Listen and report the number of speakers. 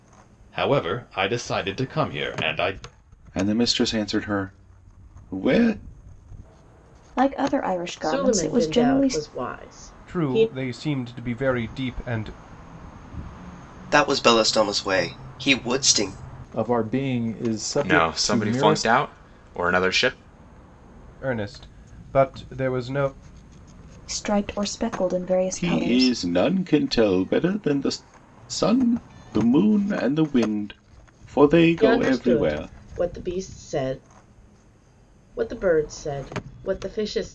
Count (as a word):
eight